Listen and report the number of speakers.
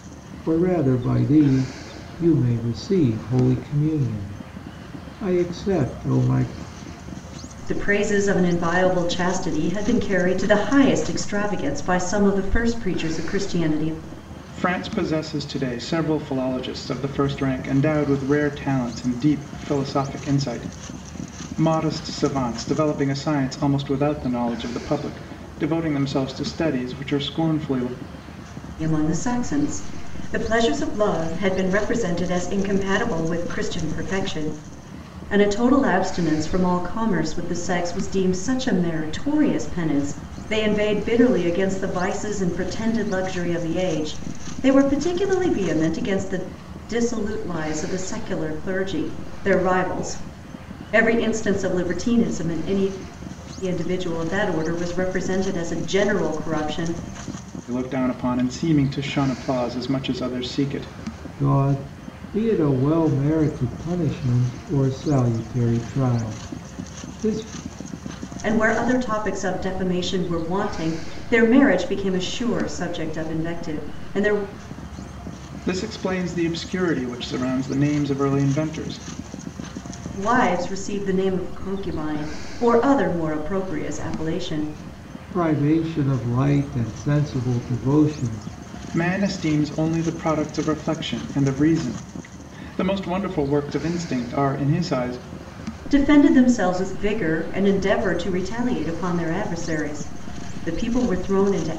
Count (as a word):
three